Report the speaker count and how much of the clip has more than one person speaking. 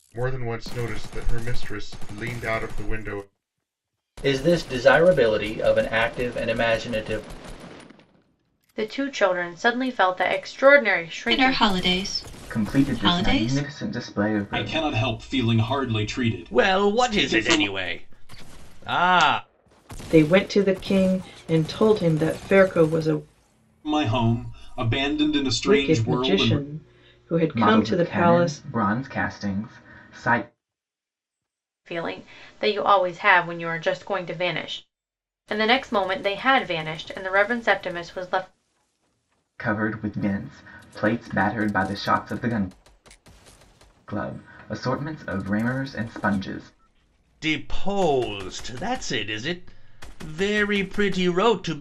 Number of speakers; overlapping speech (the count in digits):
8, about 11%